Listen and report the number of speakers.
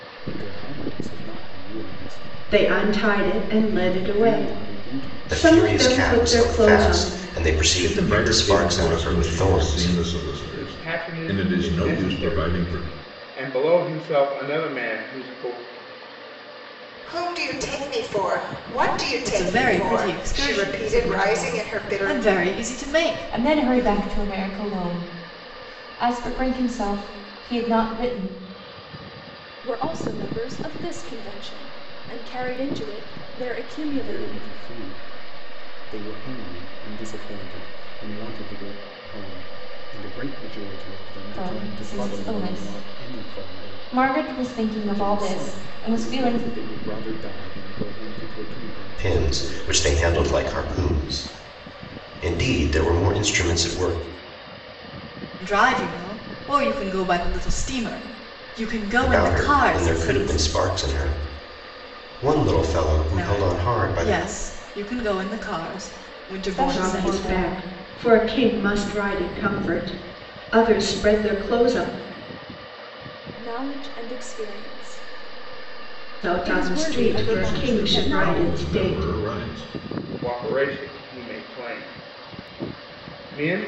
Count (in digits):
9